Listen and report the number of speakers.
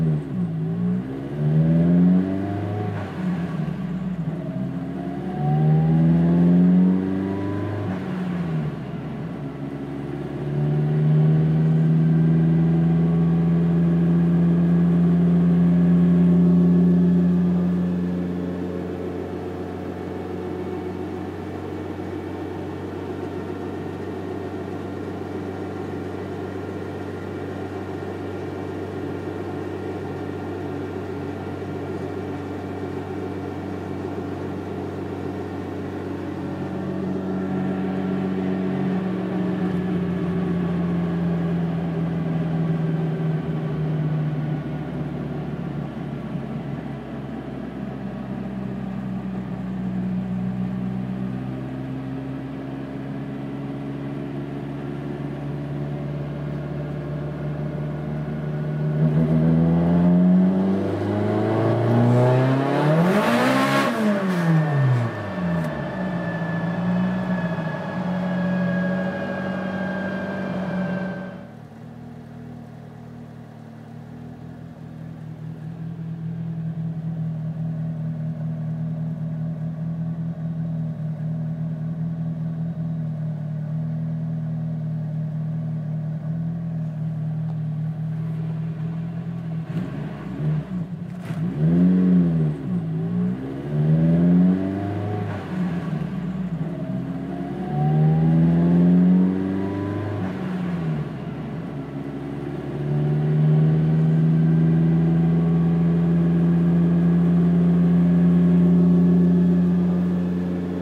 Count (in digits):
0